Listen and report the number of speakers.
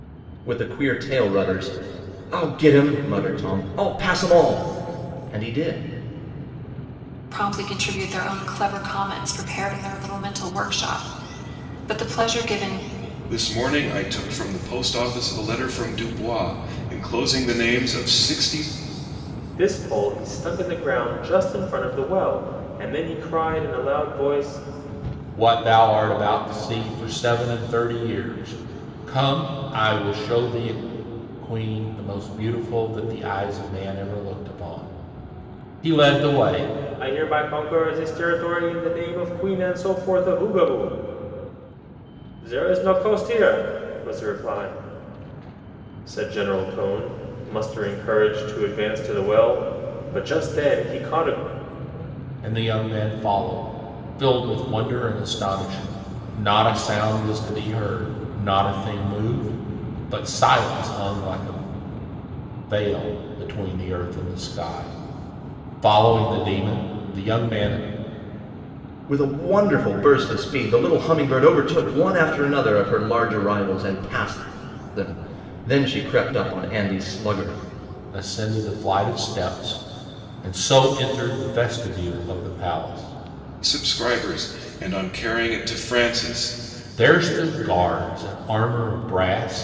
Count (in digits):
5